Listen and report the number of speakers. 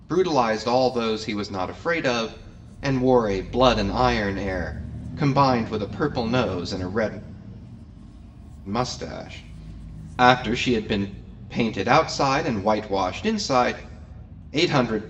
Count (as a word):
one